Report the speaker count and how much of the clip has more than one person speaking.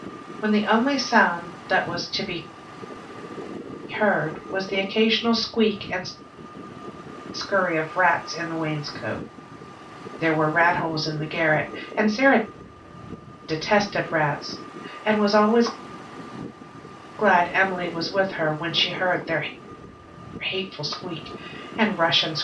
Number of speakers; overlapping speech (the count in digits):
1, no overlap